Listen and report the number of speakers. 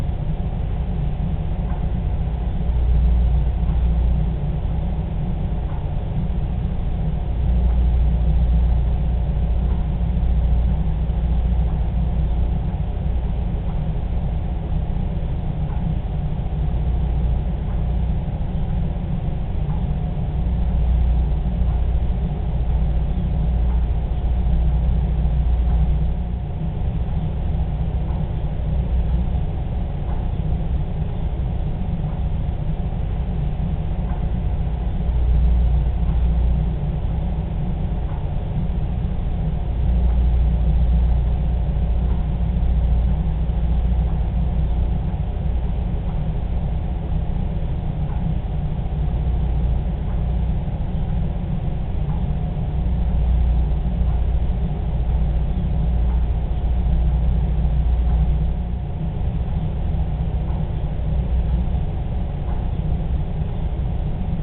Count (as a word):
zero